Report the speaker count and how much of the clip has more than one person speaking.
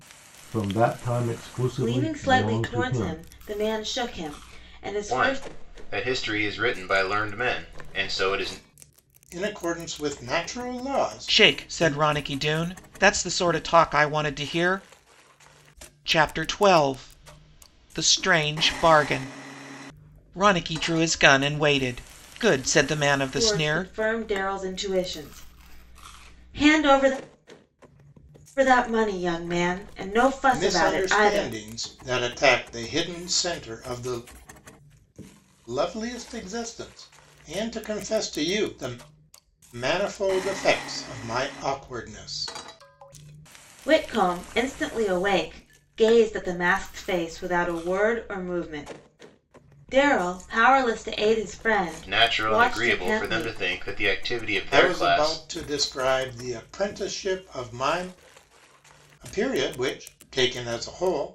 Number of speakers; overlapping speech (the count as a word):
five, about 10%